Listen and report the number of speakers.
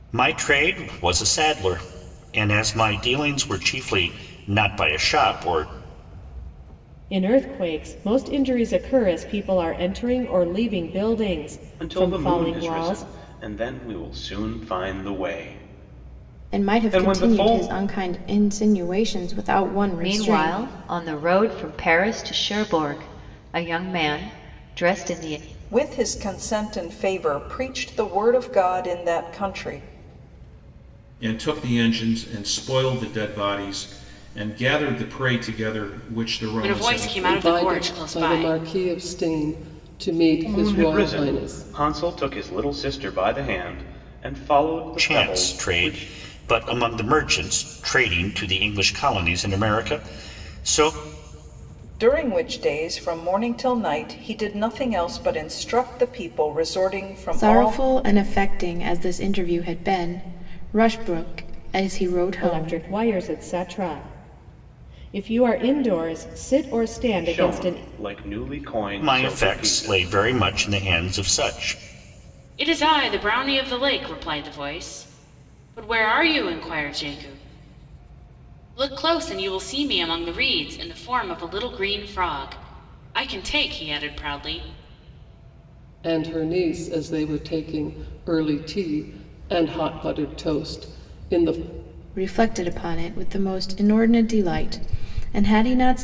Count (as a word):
nine